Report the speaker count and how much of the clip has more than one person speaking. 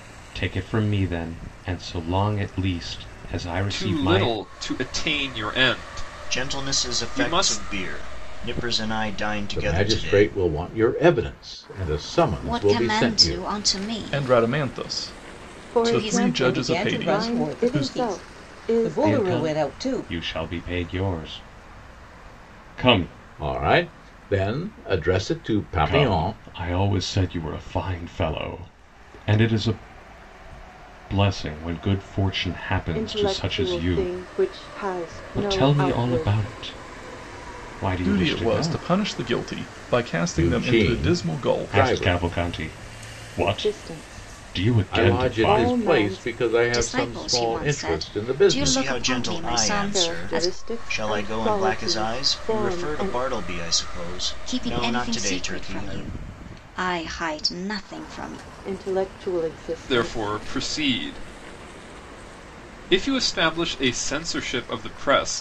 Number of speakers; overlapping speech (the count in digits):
8, about 42%